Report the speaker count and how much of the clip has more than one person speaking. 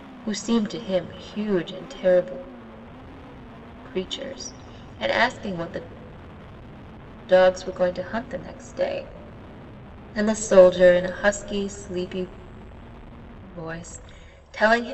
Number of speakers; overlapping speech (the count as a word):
one, no overlap